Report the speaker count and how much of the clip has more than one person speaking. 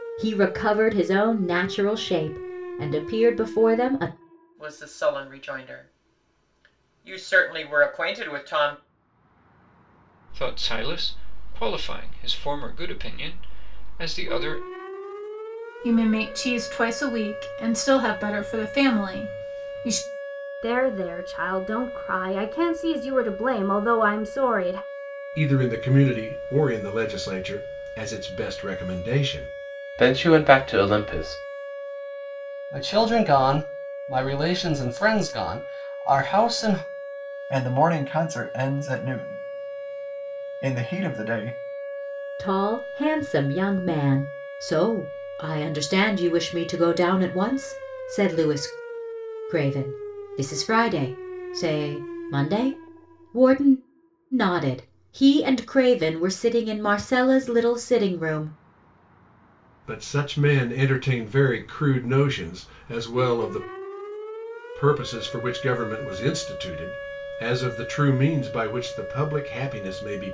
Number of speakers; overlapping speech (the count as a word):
nine, no overlap